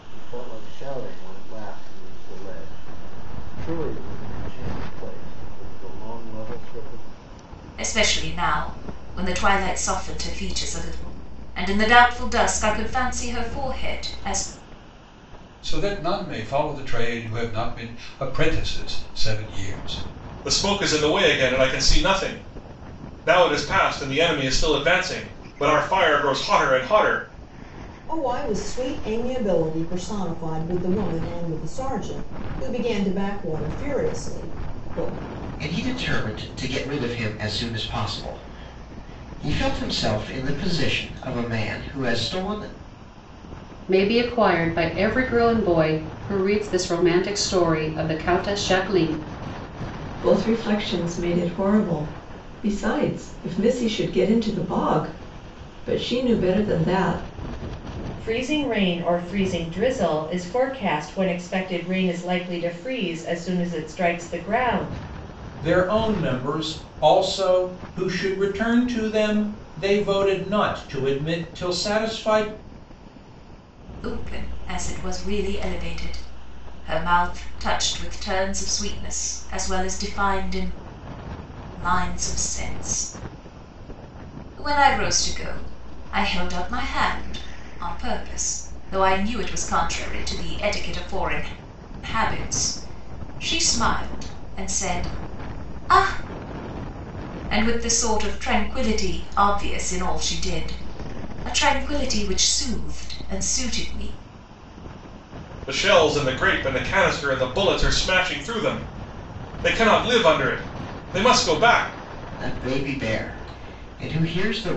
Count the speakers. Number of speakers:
10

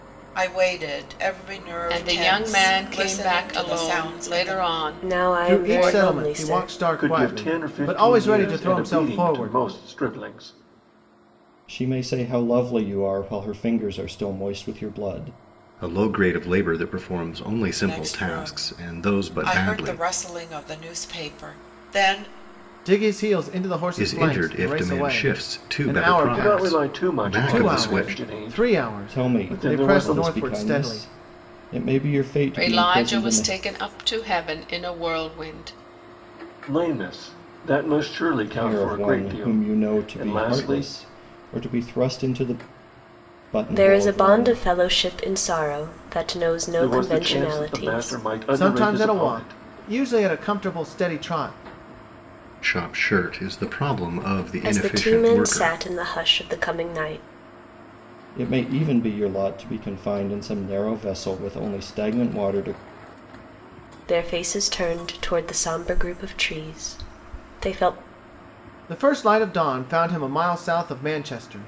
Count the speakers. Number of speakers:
7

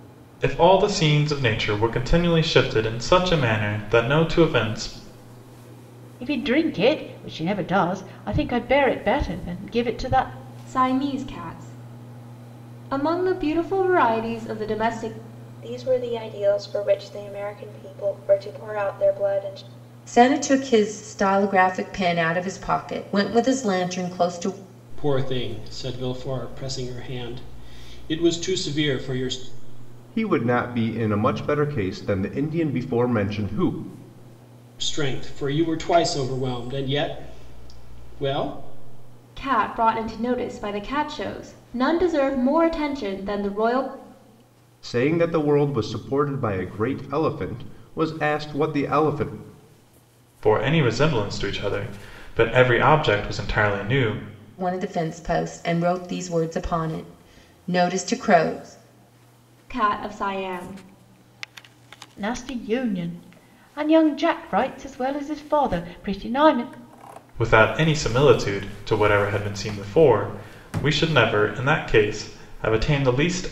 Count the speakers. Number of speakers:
7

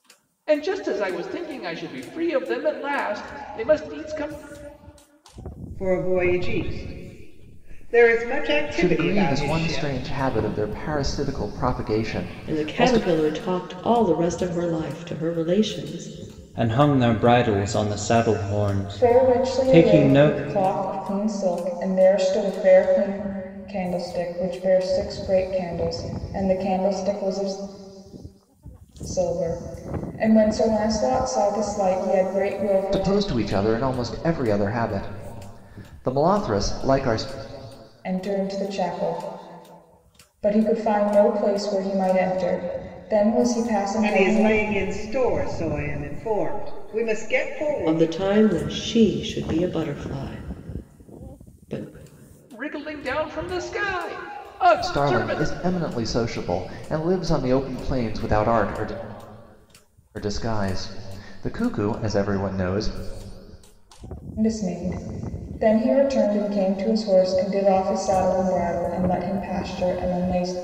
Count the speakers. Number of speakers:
6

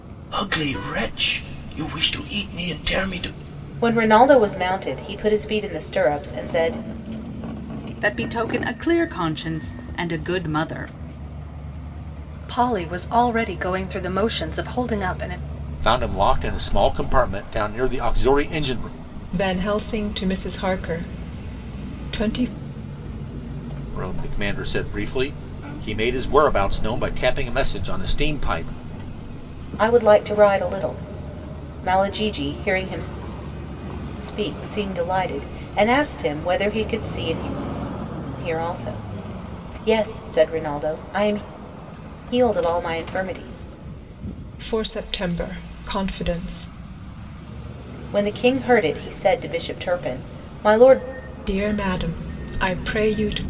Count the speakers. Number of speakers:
6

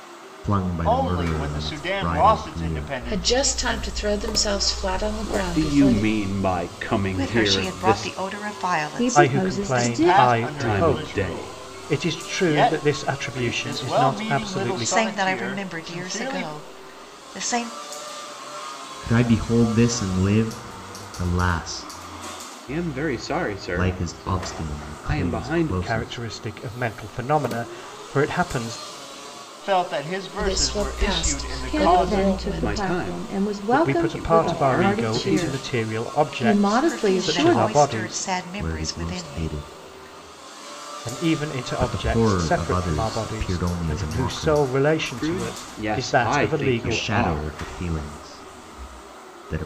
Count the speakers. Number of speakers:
7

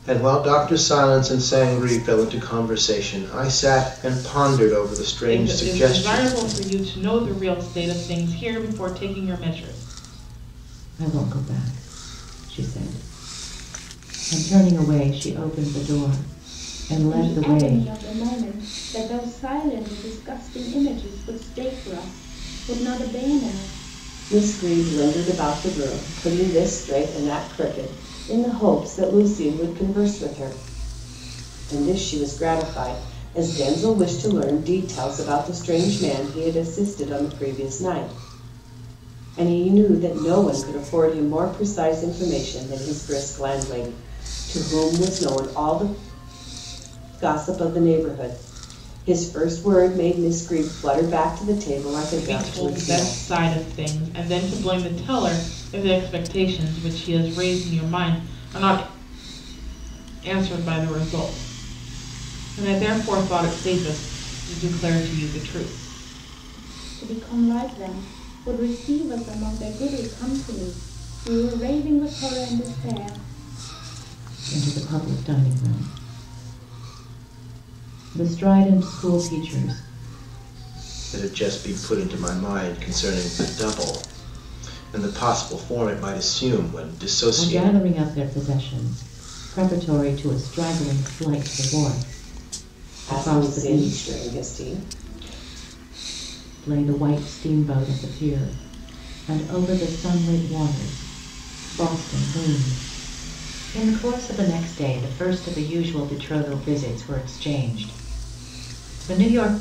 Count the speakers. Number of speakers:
5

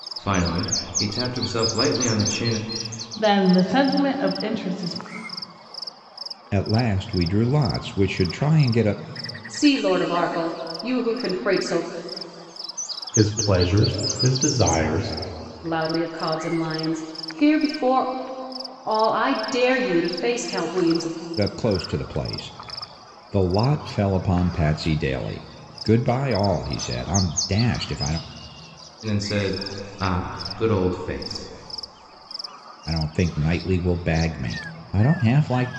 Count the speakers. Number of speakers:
5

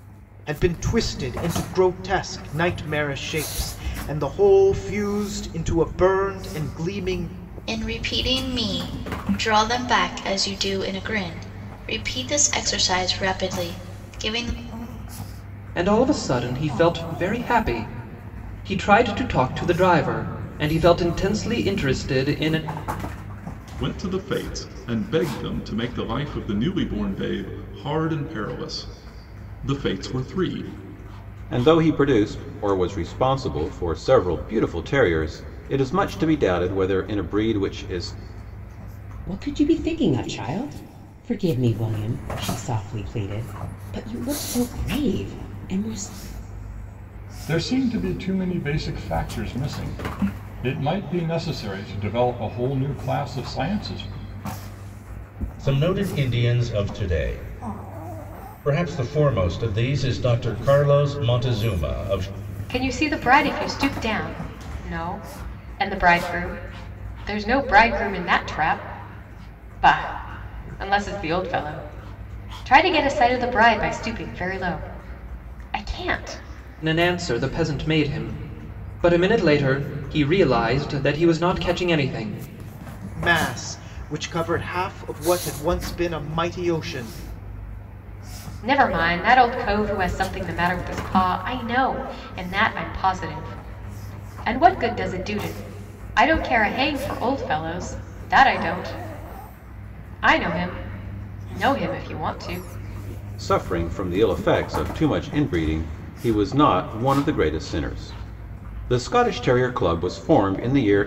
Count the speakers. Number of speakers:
9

